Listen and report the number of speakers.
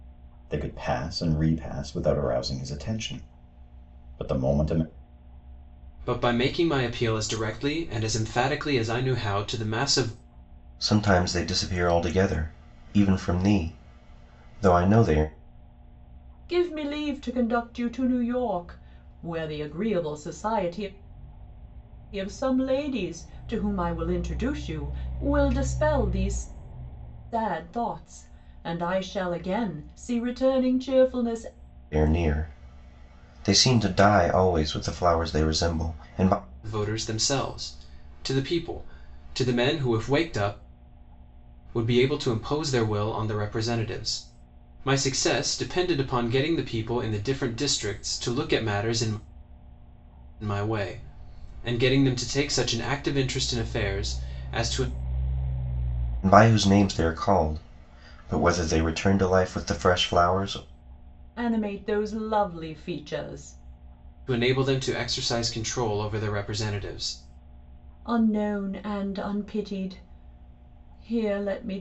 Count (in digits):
4